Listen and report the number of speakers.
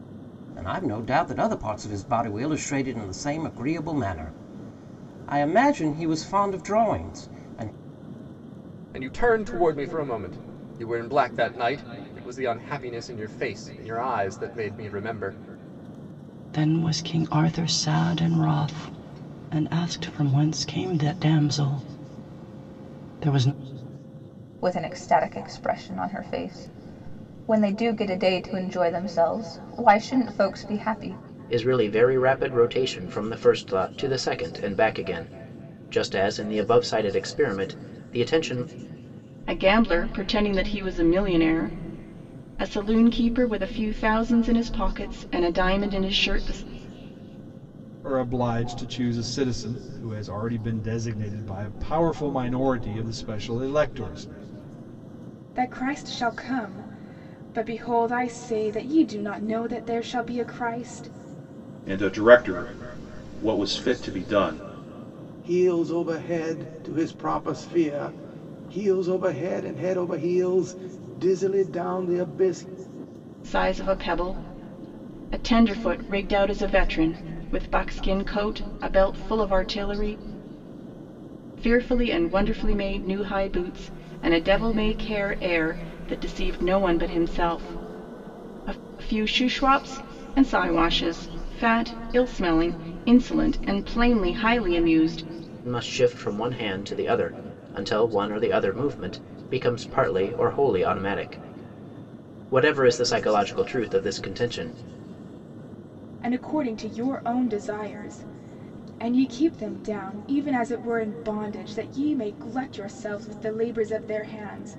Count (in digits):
10